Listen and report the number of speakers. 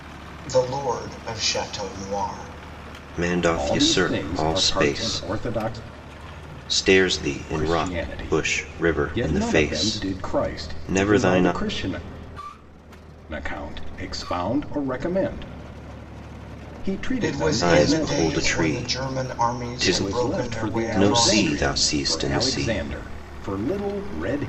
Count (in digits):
3